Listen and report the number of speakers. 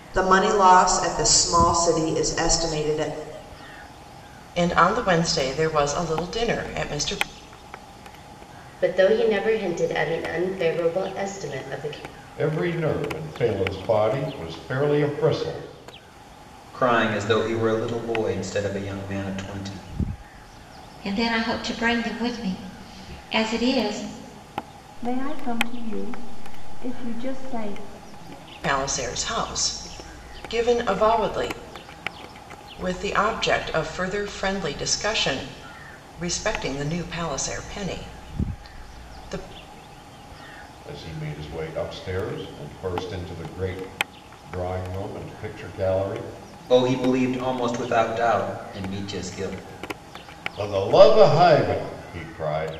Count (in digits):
7